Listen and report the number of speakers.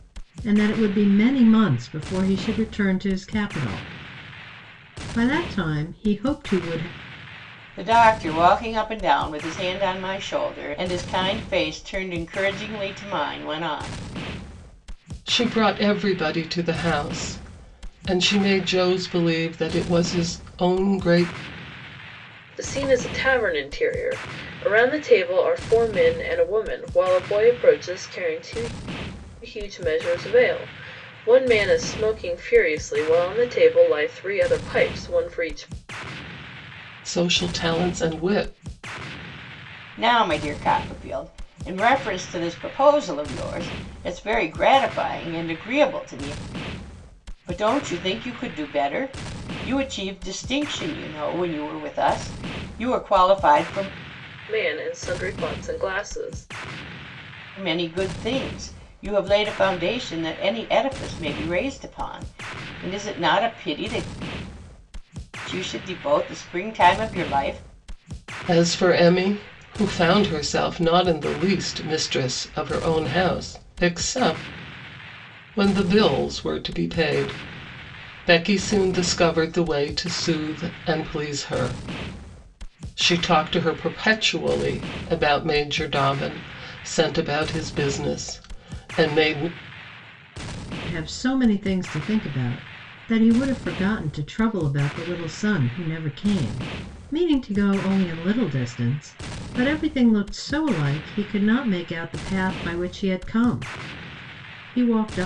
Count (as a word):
four